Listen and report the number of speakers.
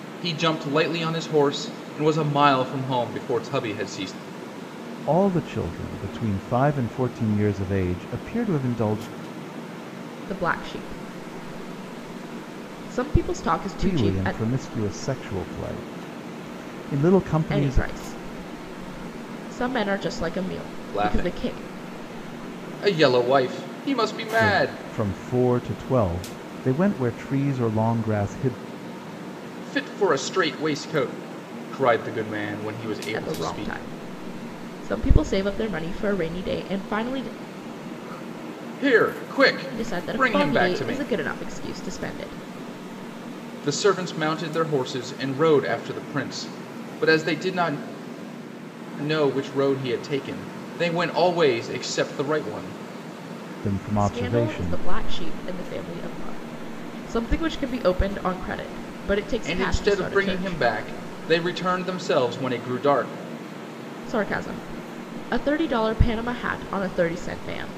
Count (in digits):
3